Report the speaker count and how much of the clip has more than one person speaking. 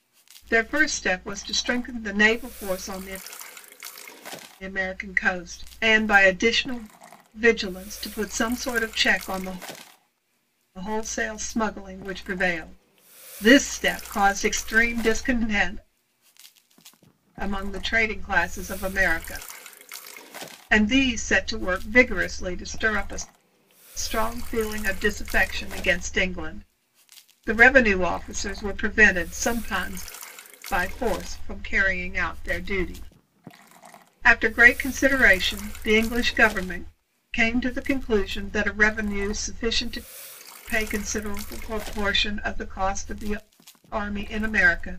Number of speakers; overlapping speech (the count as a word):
one, no overlap